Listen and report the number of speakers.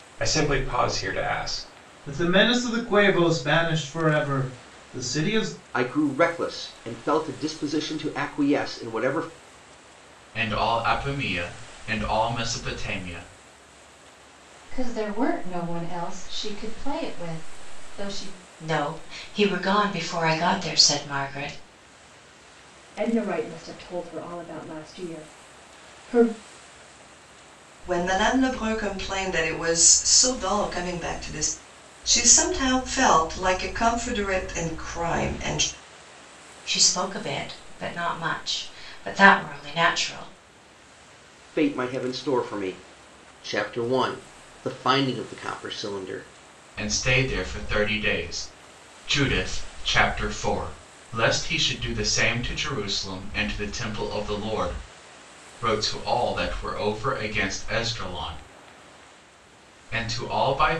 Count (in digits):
8